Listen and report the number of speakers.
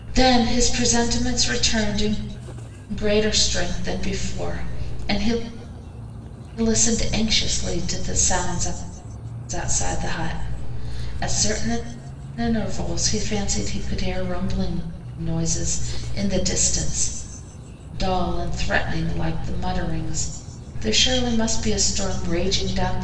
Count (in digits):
1